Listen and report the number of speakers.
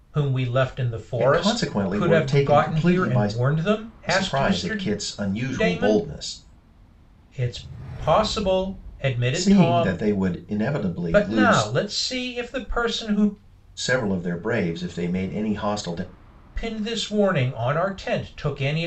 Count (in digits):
2